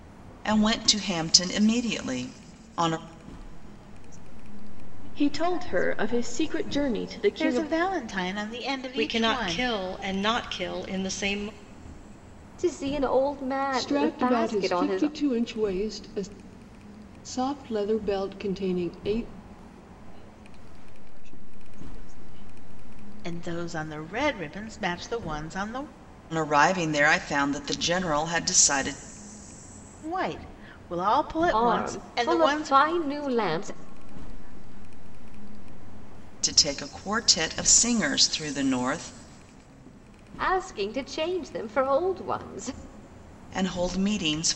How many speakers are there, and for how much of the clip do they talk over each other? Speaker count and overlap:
7, about 12%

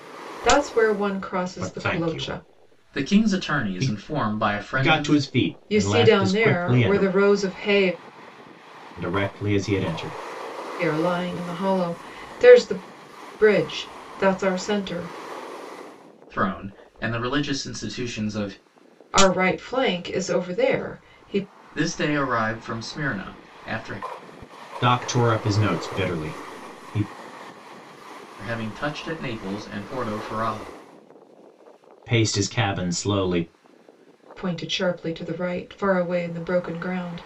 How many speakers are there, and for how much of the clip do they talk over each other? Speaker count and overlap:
3, about 10%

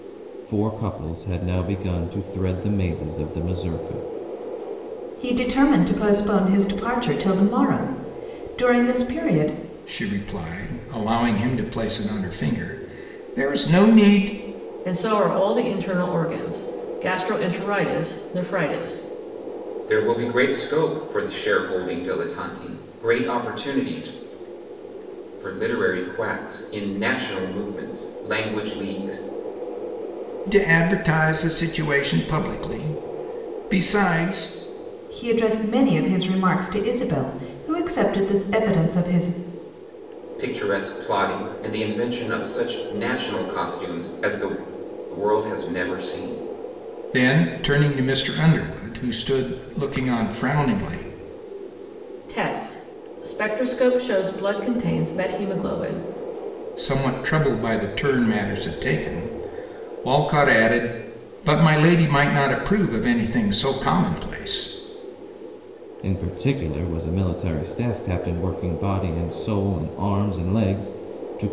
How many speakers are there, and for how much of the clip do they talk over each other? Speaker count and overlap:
5, no overlap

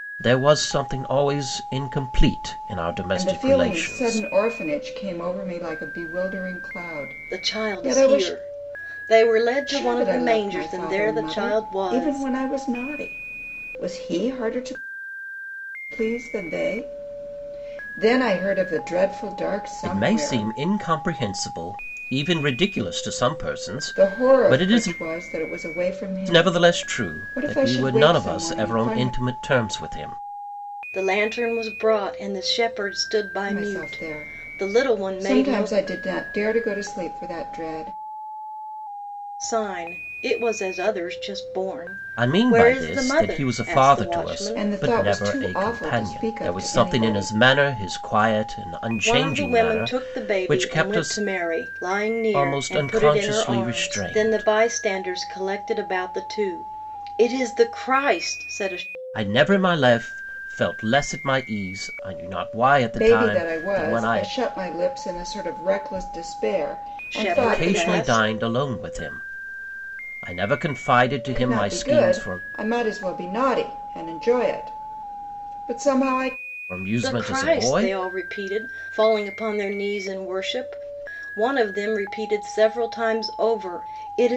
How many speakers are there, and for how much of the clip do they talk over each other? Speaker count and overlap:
3, about 31%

